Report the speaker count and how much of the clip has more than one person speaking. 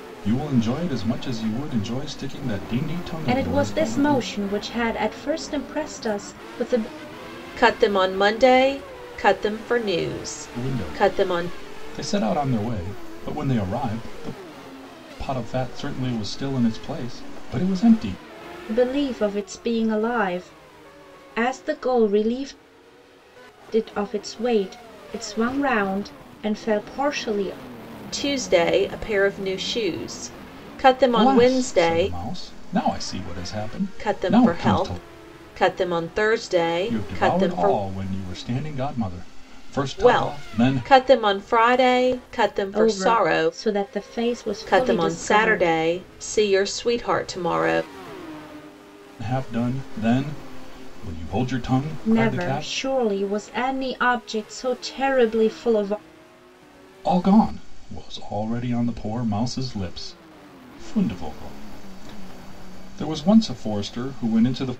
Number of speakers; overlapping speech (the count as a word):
three, about 13%